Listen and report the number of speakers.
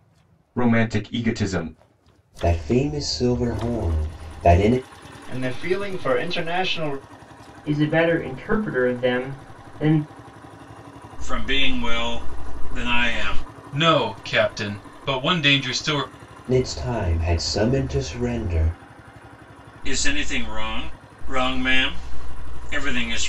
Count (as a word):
six